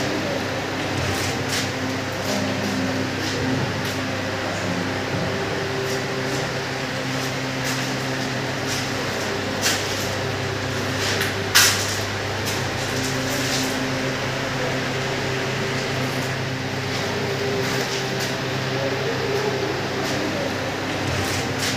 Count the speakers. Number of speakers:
0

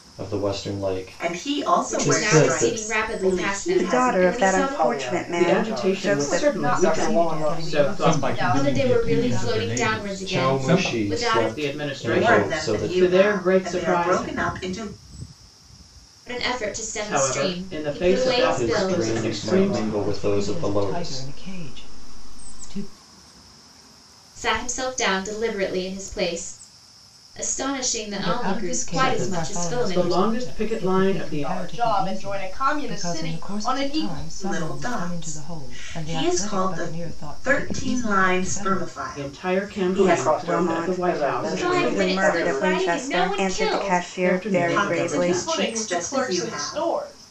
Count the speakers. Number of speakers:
9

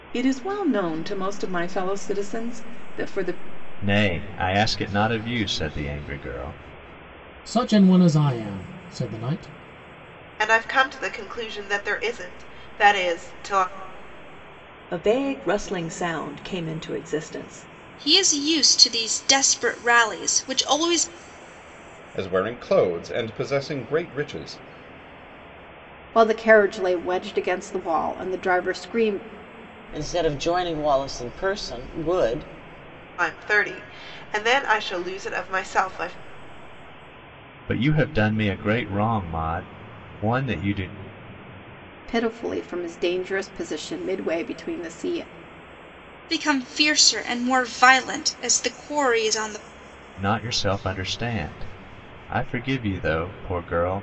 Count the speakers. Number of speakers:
9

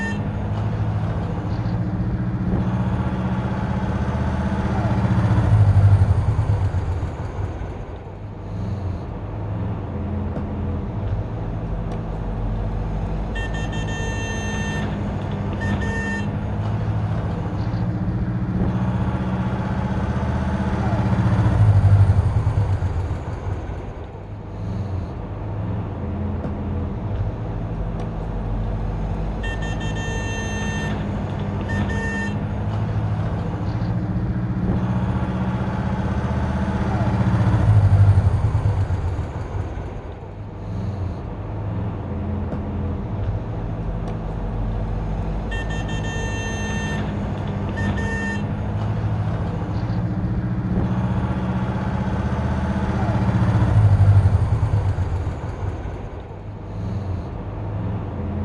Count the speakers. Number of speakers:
0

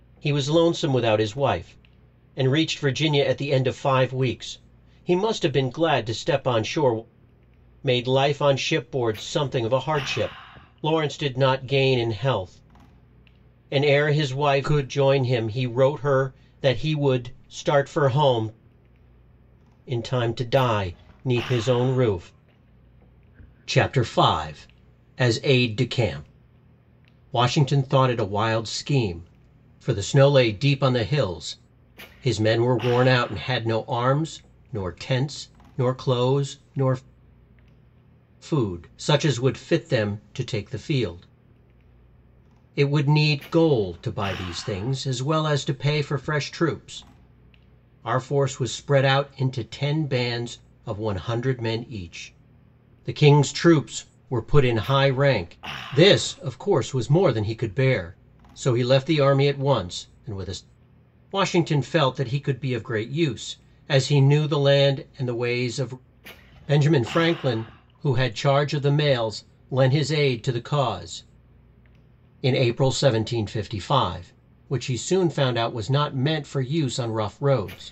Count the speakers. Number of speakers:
1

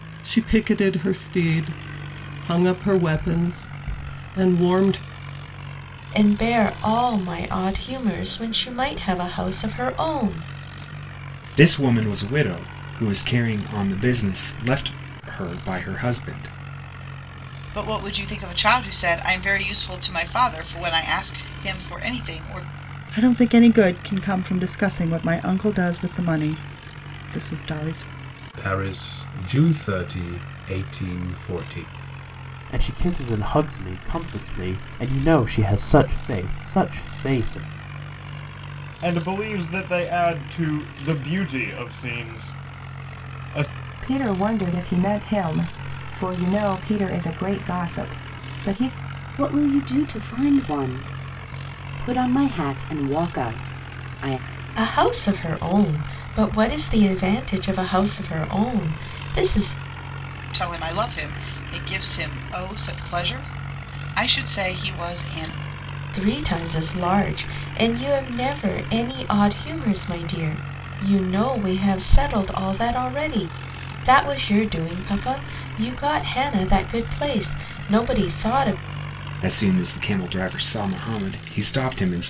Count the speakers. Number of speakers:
10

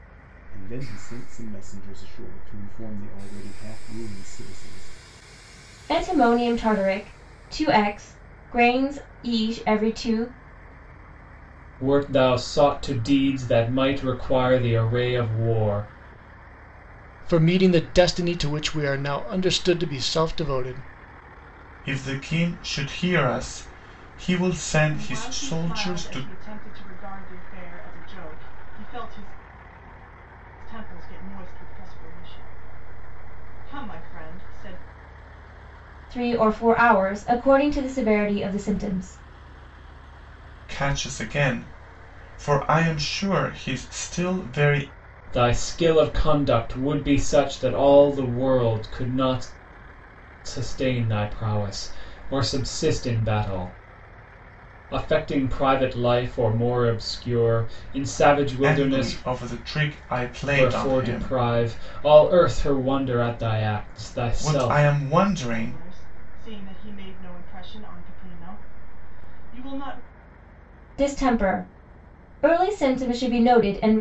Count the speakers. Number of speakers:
6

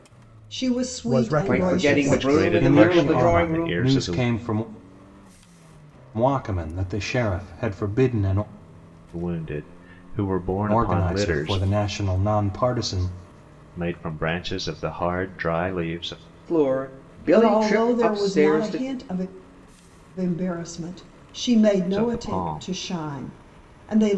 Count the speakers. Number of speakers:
5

